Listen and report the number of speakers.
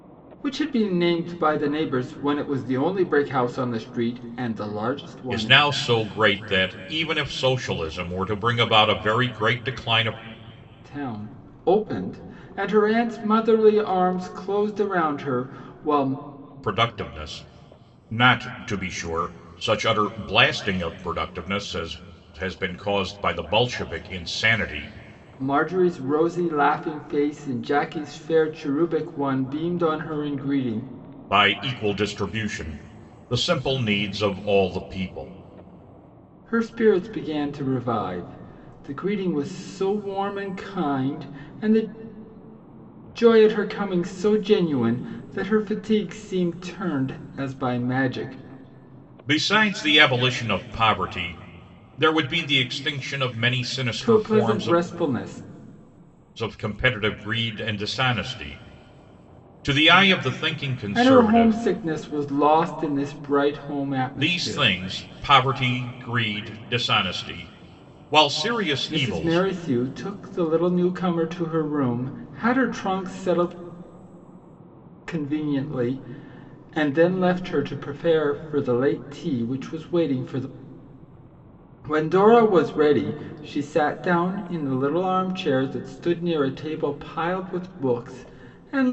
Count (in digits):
2